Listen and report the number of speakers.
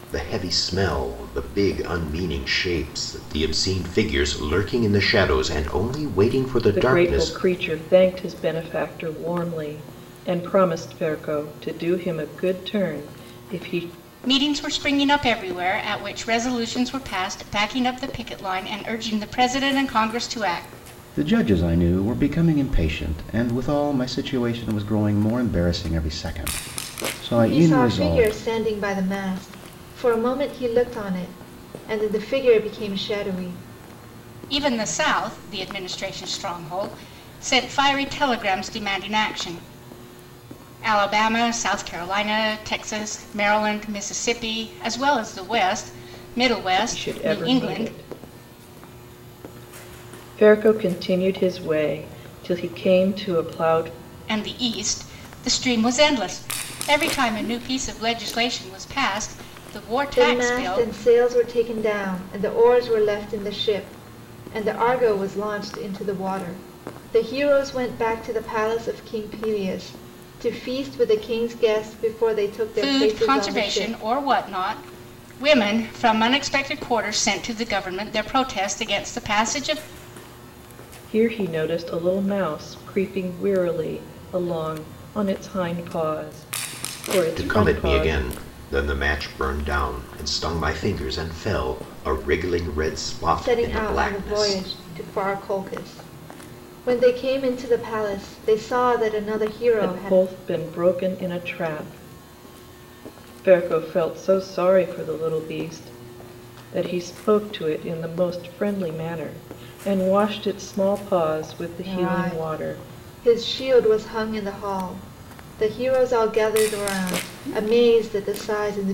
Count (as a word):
five